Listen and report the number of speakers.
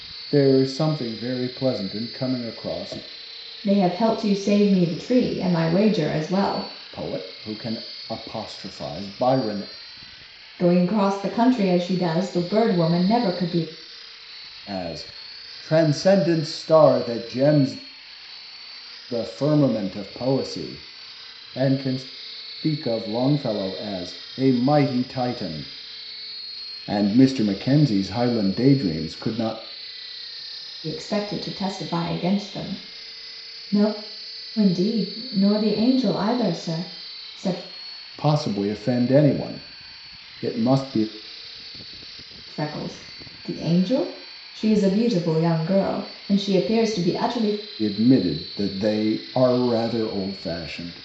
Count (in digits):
2